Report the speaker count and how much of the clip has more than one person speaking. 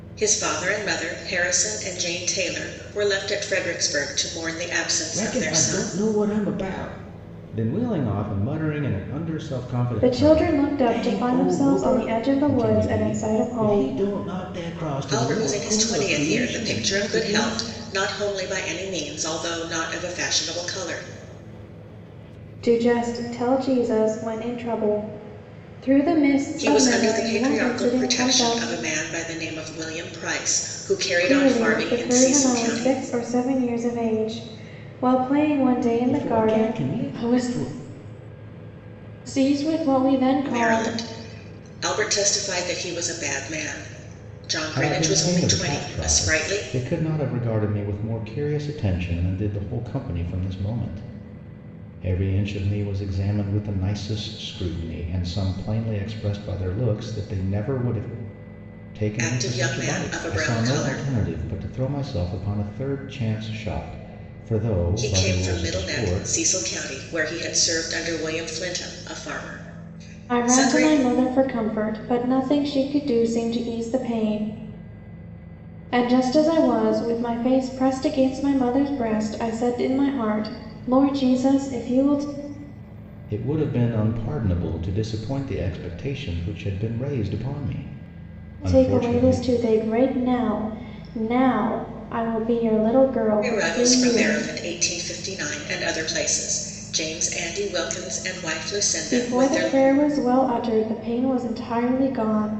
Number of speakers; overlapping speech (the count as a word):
three, about 21%